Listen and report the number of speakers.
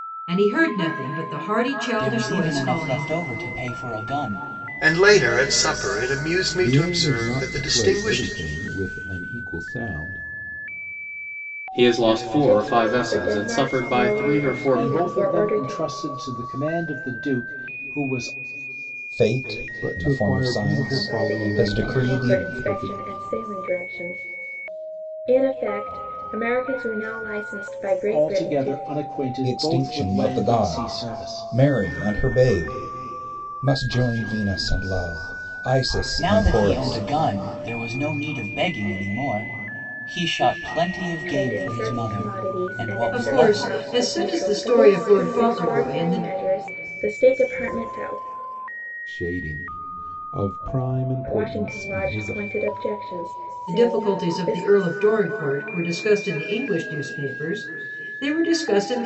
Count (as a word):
eight